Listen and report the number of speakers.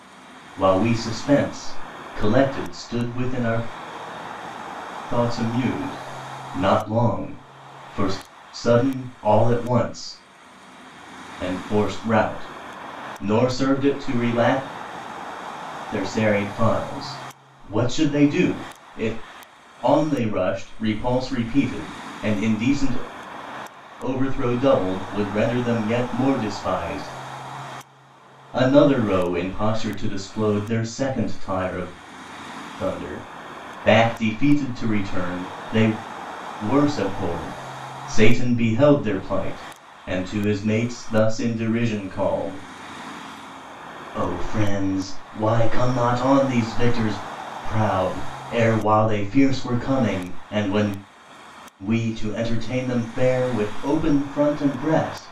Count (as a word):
one